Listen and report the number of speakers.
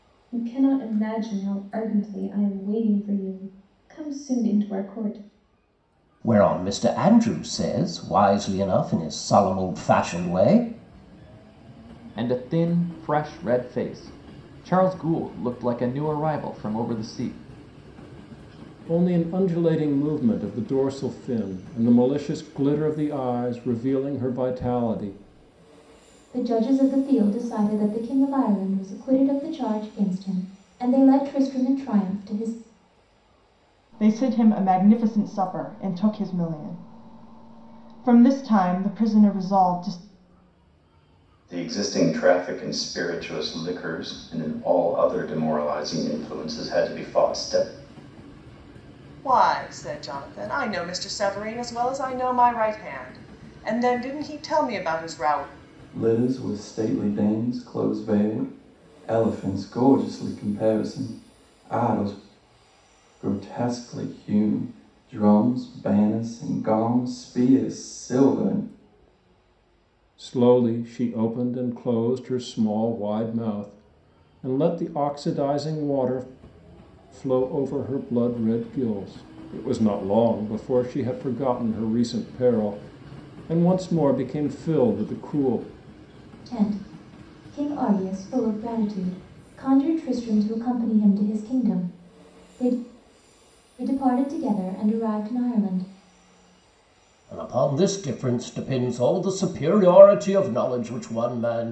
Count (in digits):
9